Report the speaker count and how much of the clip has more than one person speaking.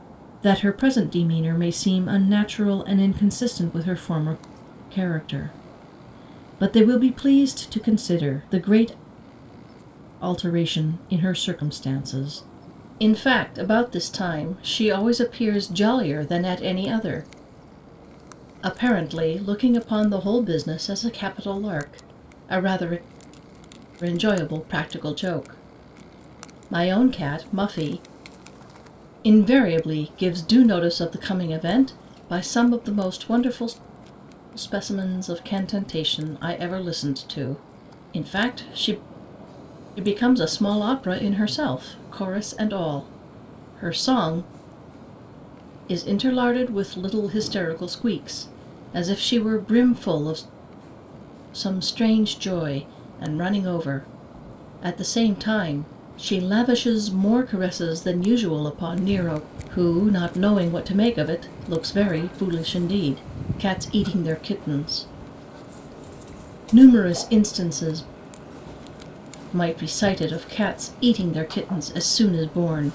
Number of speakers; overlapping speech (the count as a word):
one, no overlap